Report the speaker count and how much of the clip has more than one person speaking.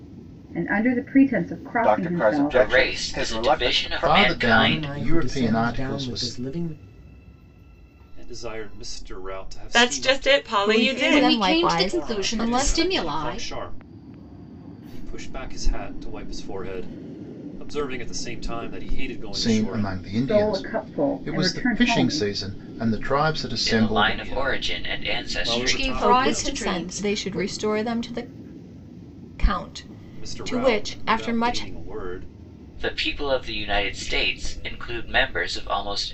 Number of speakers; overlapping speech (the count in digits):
9, about 45%